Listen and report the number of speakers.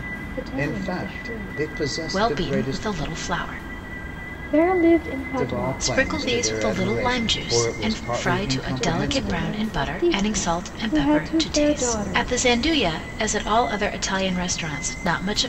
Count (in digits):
3